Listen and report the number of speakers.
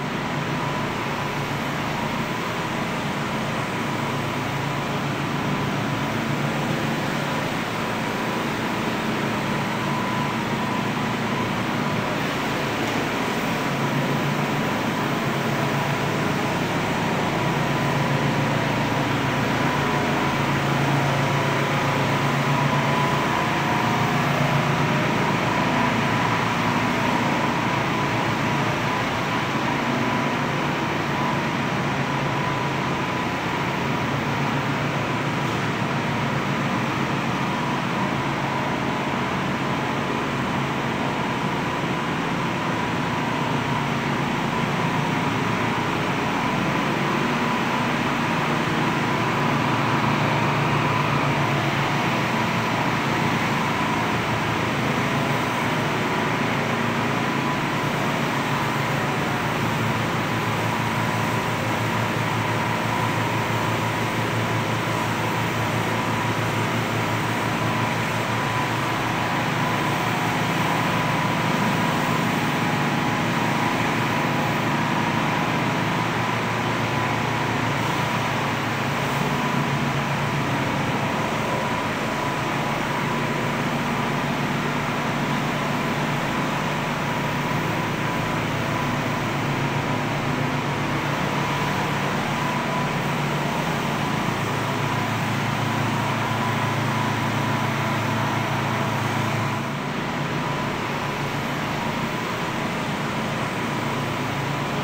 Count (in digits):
0